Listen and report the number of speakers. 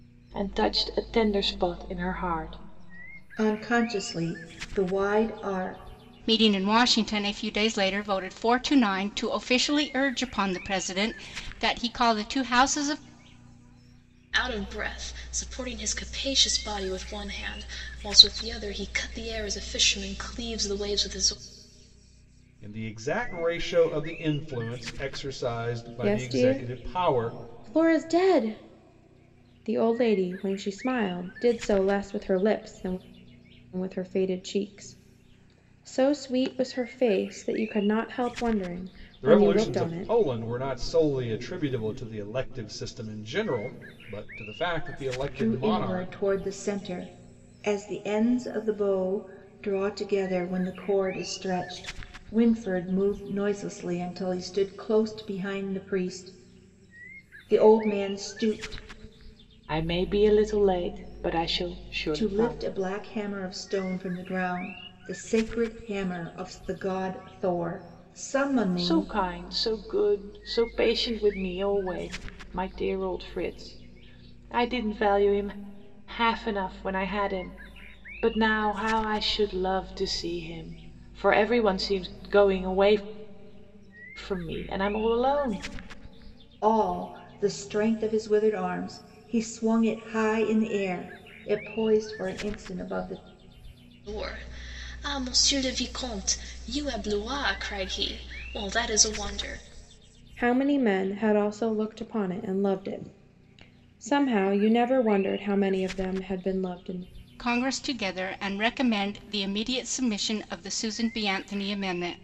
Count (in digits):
6